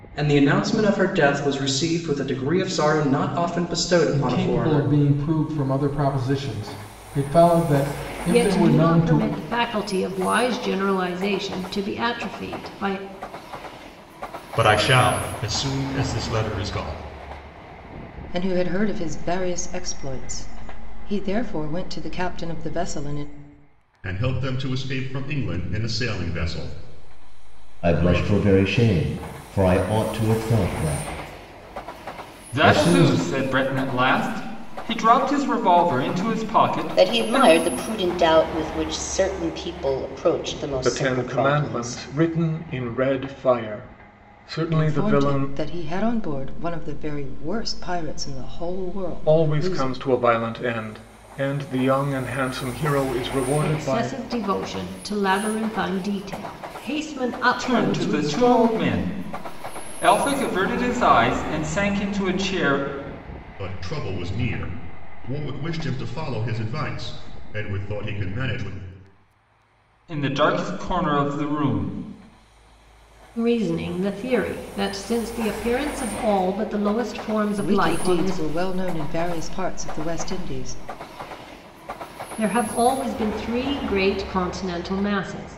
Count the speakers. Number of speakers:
10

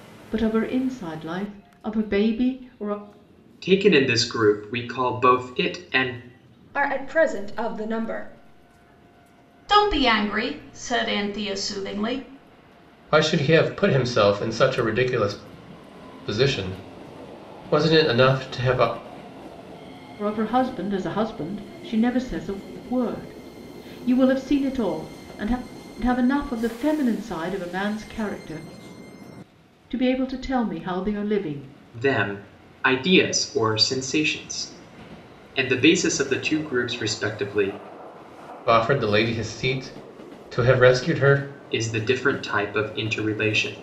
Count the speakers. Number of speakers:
5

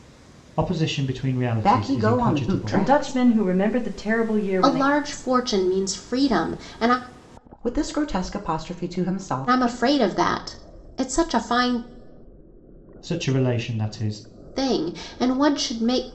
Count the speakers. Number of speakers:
4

